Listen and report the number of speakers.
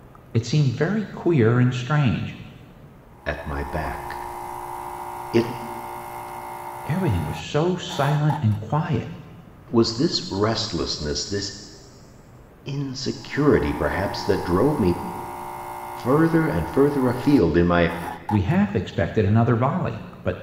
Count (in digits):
2